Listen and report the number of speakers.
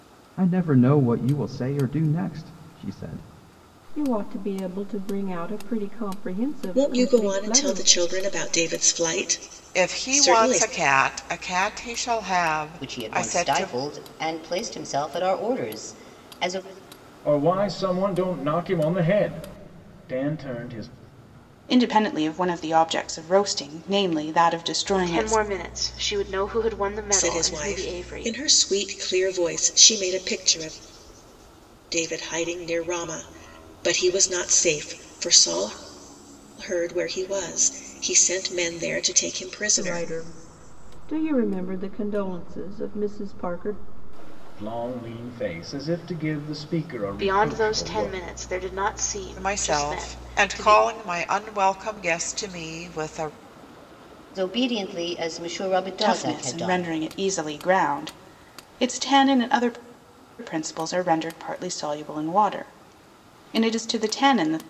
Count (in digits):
8